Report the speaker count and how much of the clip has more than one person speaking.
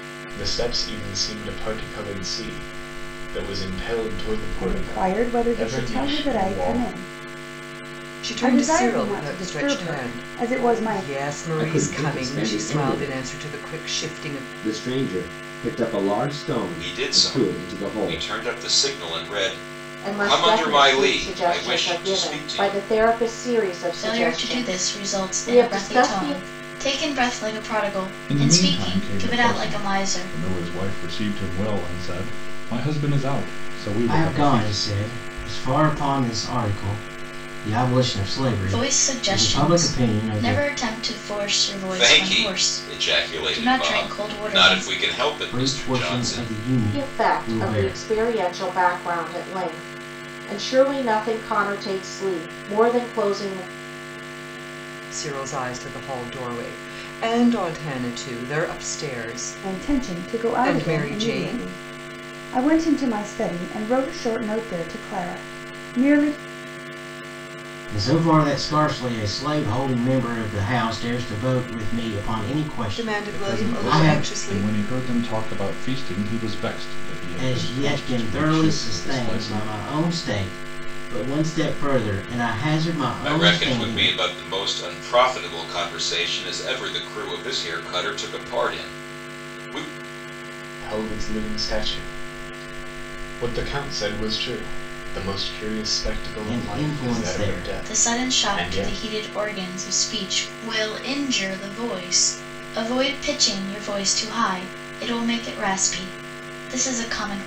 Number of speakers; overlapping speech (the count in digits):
9, about 32%